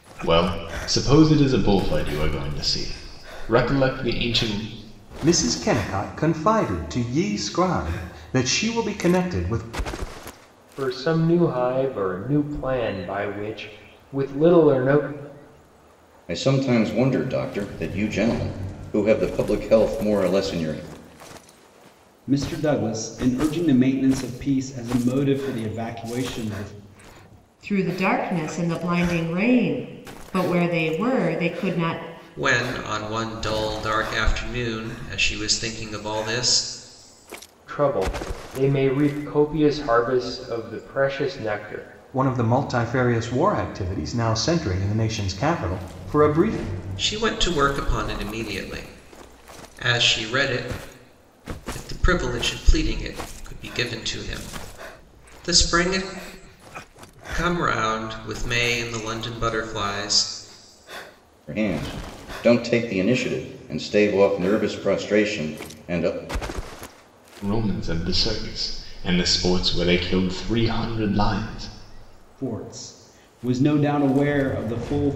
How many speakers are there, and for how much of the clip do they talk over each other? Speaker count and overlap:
7, no overlap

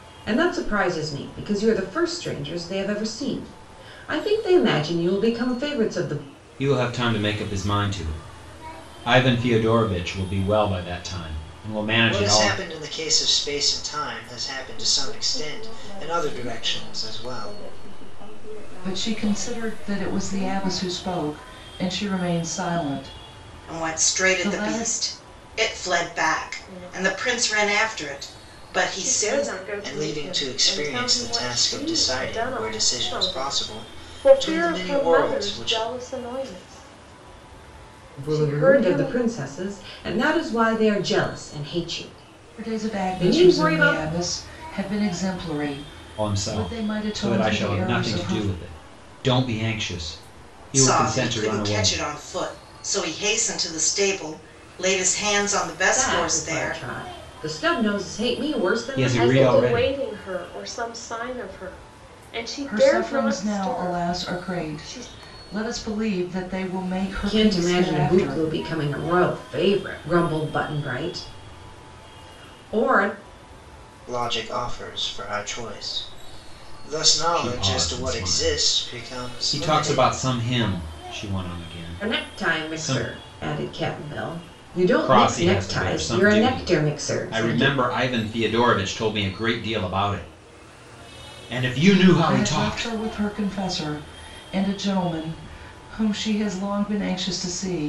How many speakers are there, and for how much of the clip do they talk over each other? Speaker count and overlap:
7, about 35%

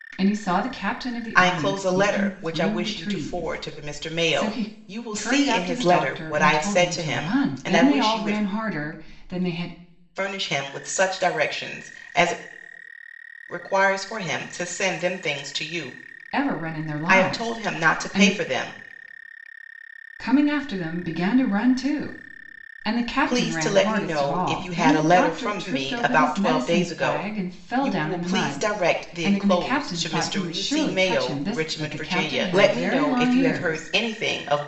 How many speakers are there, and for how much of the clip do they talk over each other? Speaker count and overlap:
2, about 54%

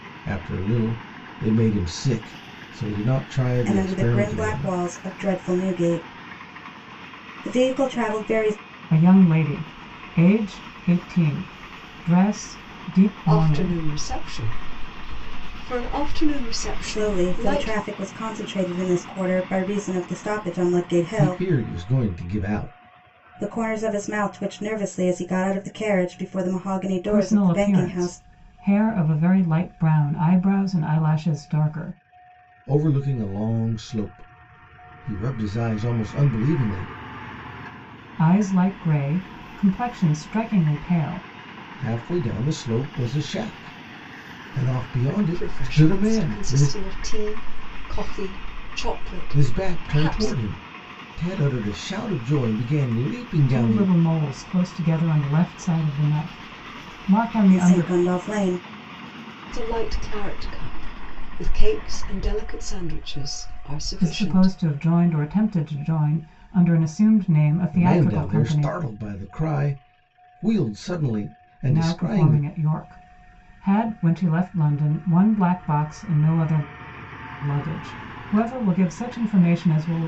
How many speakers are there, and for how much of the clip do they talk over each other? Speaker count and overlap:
4, about 12%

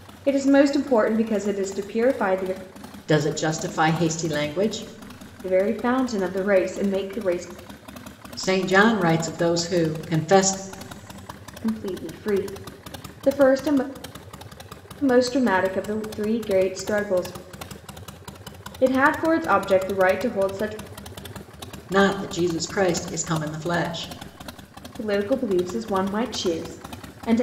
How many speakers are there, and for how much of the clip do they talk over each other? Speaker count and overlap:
2, no overlap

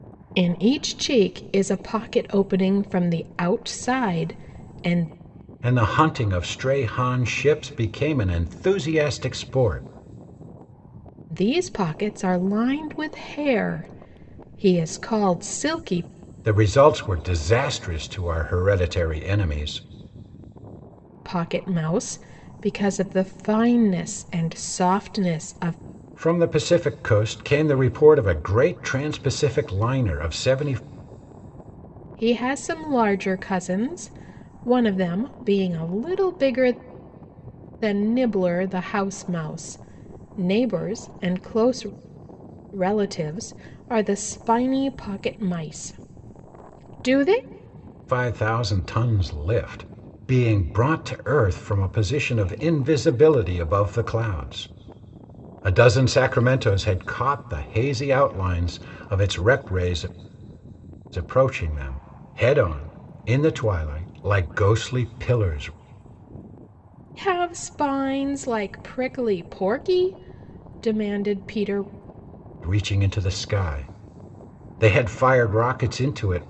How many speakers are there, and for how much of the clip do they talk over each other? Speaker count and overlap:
2, no overlap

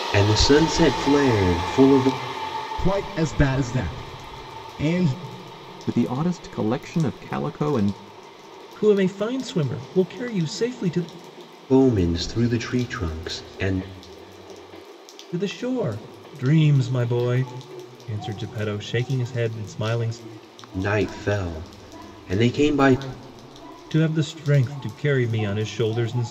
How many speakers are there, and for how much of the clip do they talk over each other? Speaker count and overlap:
4, no overlap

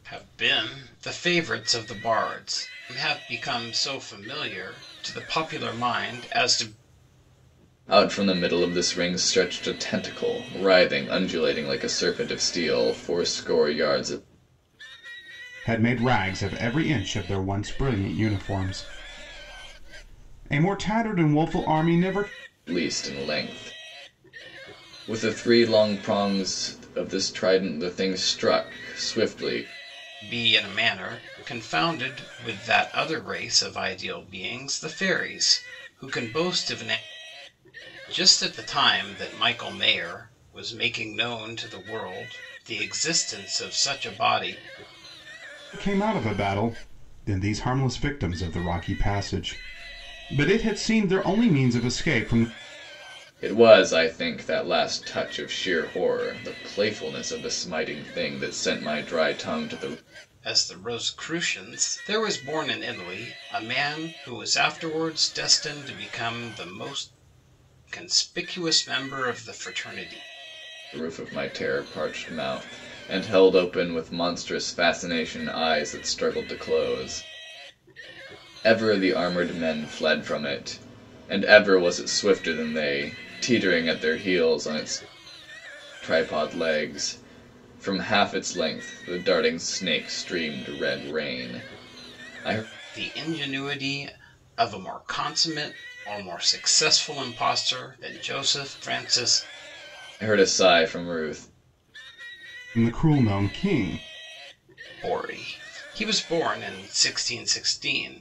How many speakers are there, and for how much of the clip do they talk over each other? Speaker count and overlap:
3, no overlap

